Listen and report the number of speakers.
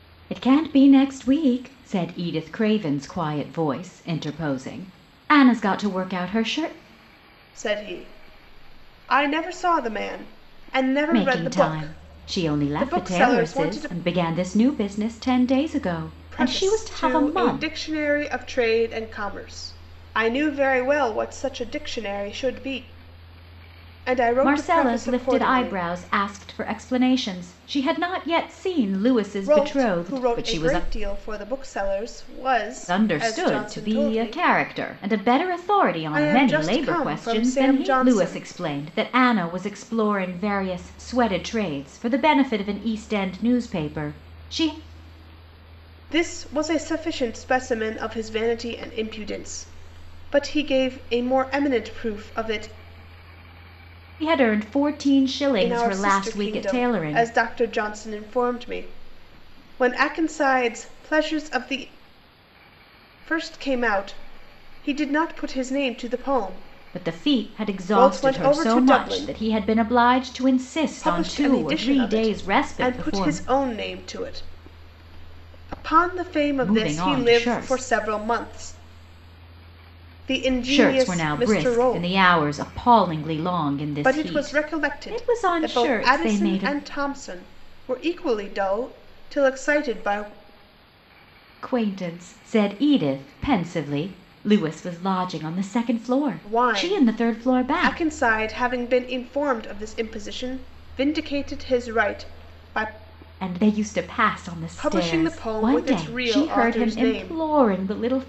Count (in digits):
2